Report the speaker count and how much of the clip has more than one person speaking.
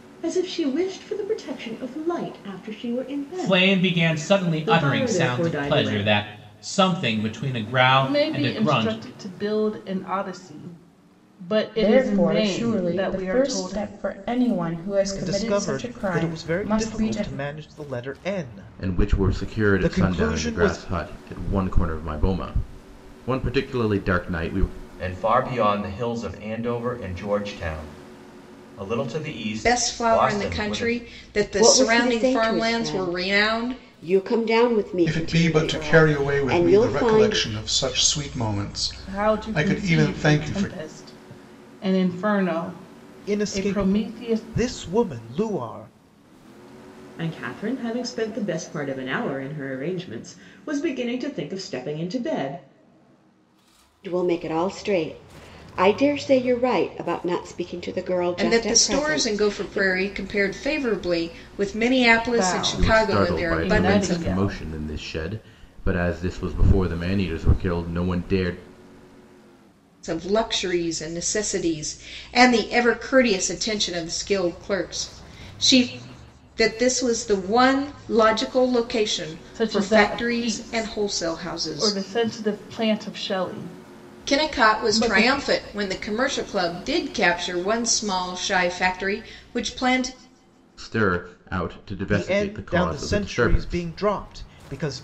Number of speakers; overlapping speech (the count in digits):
10, about 30%